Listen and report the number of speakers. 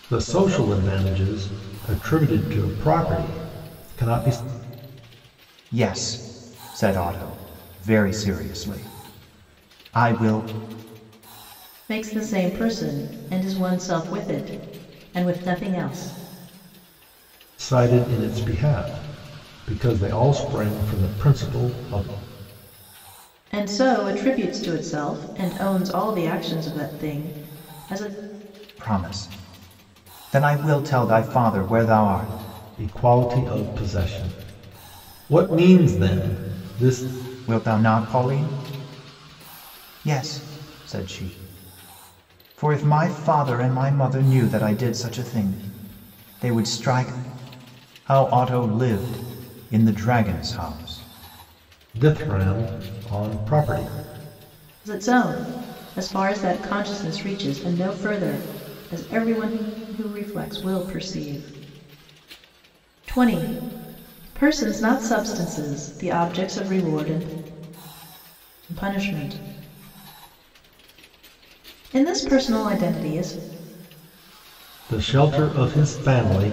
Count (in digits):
3